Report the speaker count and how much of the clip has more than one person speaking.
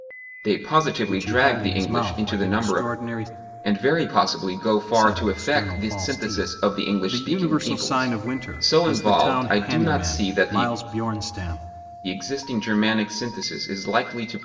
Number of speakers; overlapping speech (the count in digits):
2, about 49%